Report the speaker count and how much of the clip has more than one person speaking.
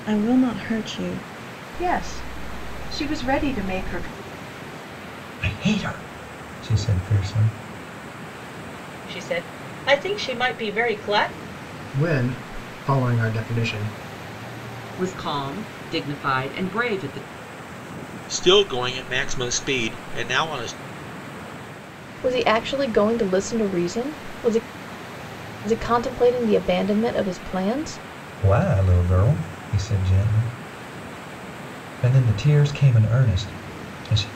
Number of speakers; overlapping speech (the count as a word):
eight, no overlap